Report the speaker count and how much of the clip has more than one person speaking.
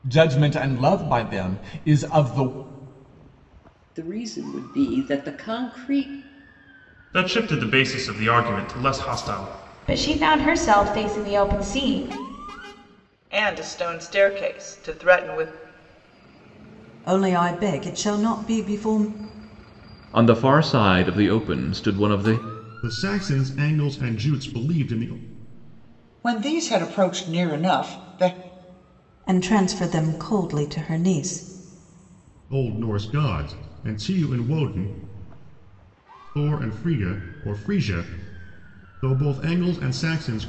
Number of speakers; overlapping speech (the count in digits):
9, no overlap